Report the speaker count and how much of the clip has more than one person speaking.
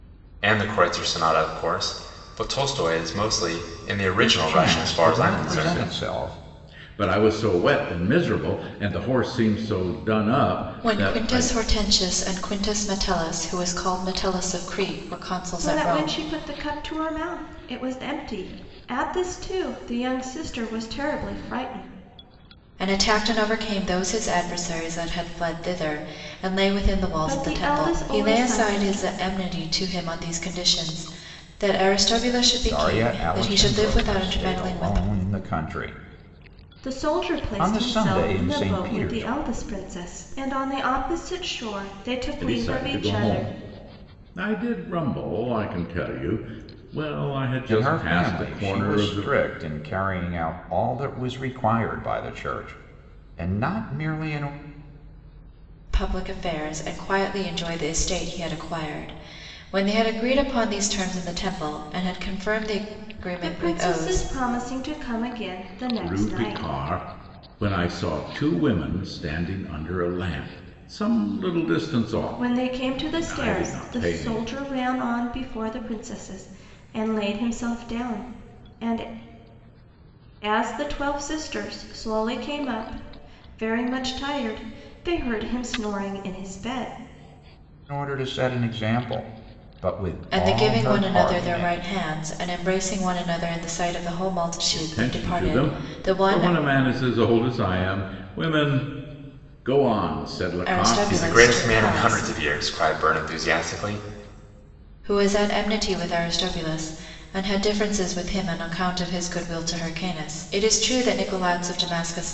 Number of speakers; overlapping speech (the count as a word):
five, about 20%